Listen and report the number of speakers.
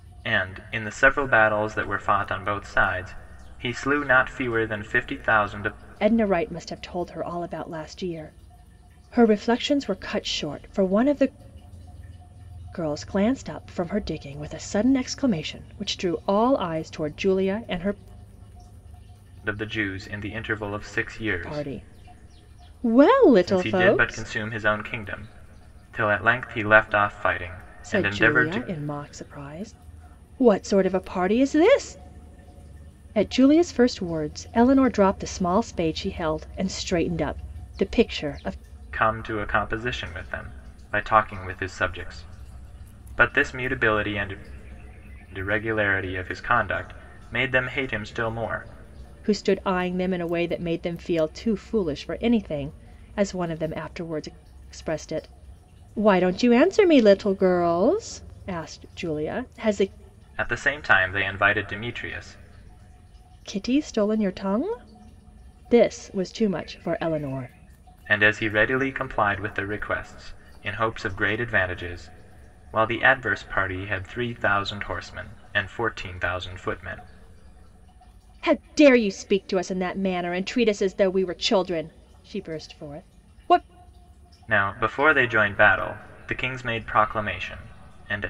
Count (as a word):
two